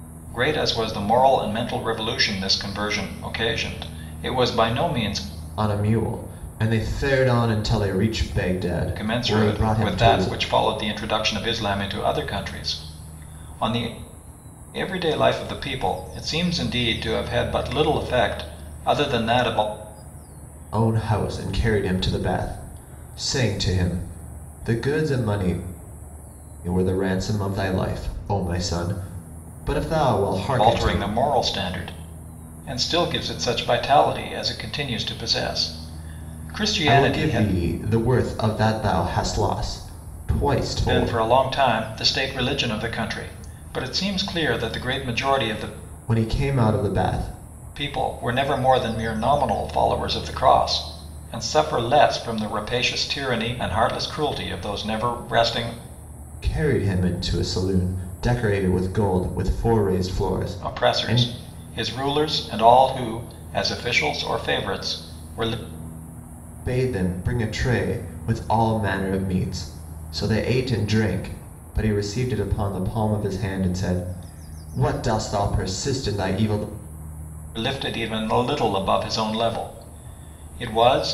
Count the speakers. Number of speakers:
2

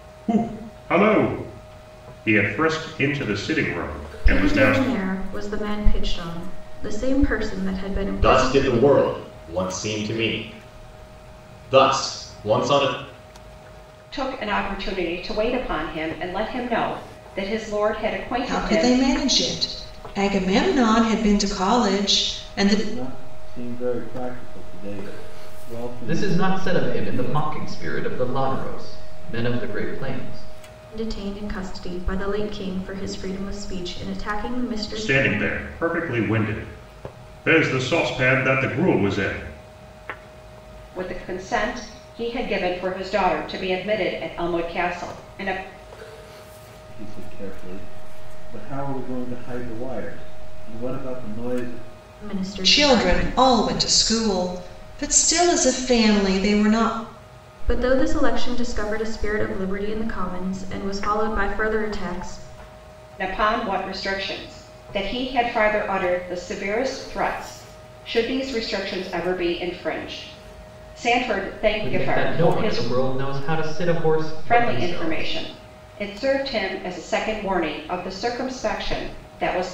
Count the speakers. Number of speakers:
7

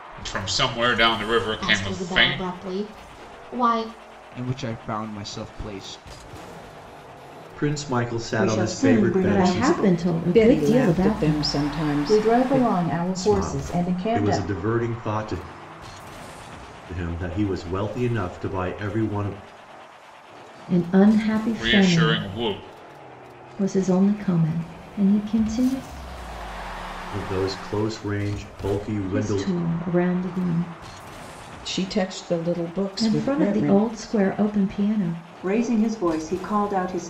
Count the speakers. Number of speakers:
8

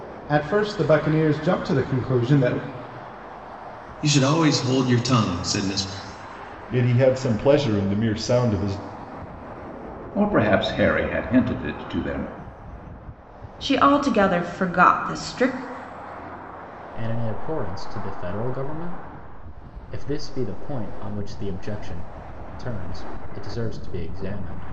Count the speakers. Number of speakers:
6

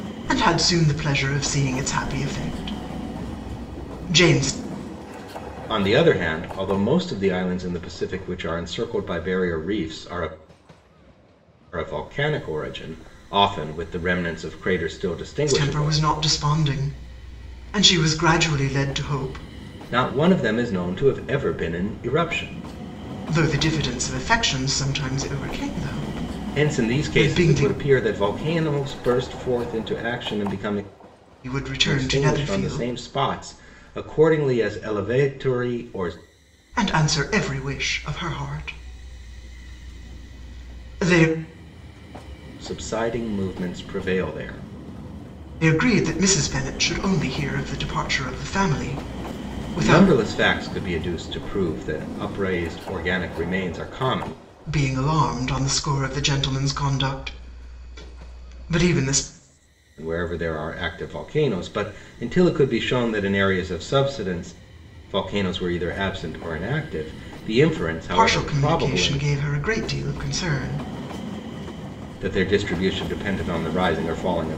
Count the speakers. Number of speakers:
2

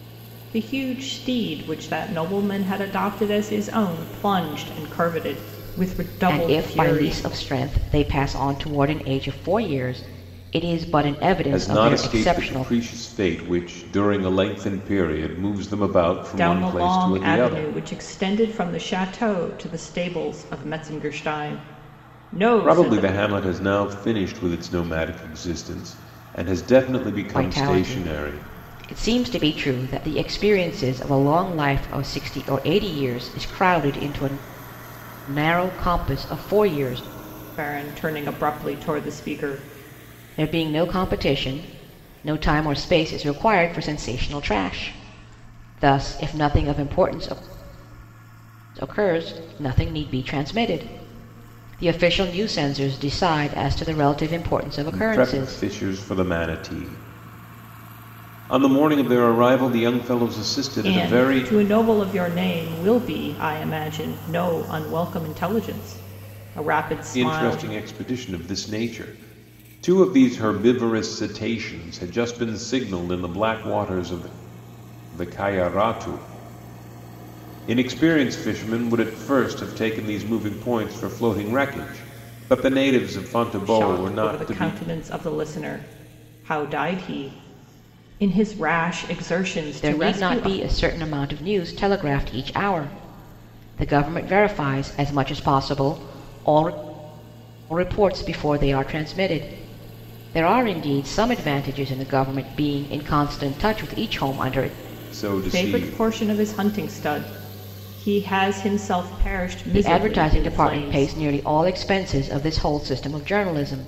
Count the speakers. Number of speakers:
3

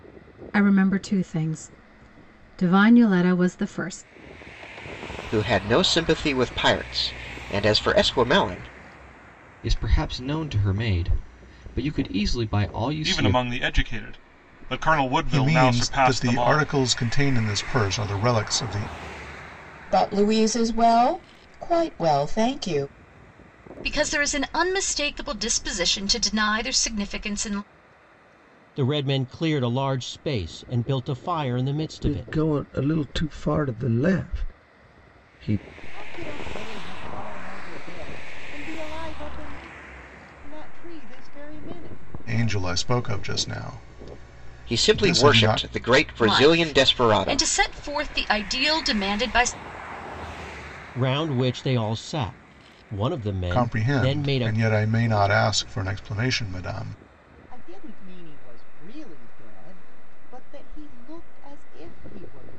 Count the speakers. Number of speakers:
10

